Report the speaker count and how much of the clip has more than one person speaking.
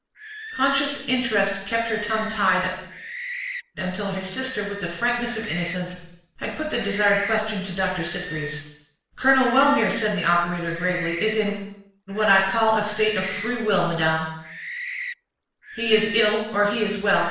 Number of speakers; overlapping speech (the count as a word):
one, no overlap